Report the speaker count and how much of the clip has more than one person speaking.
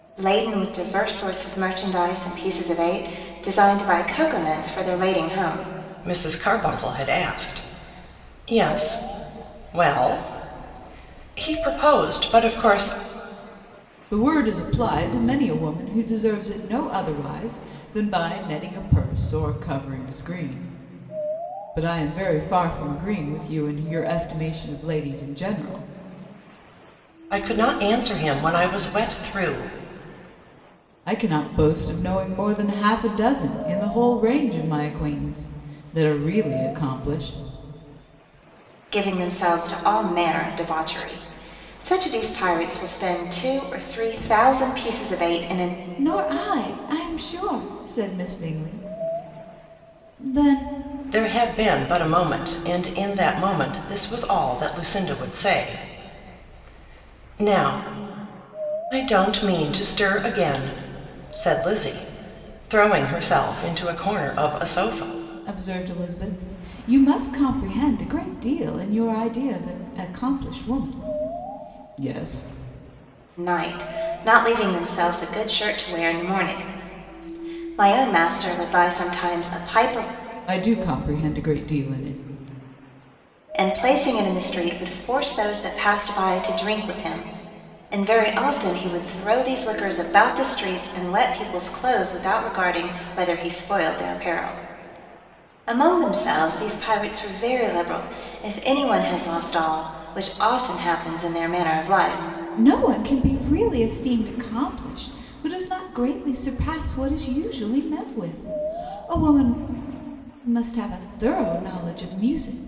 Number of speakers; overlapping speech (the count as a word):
three, no overlap